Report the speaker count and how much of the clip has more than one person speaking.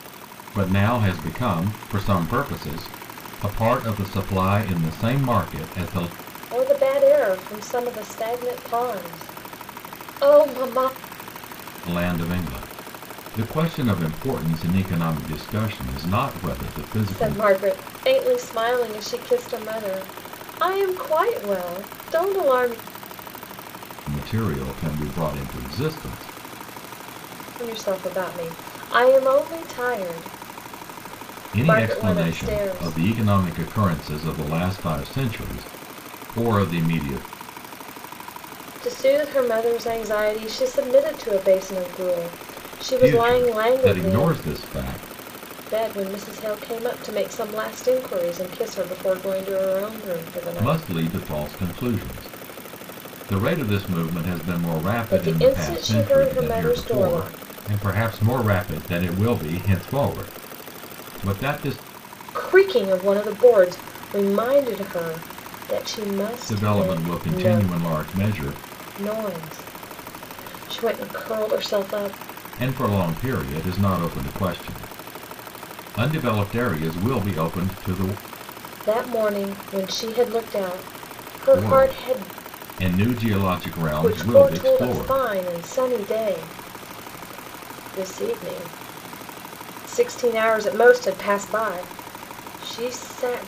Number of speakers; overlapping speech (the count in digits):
2, about 10%